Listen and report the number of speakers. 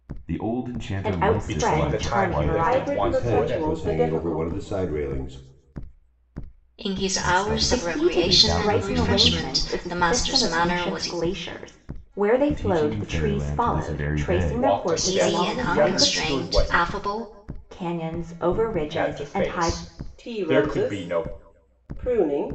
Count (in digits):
6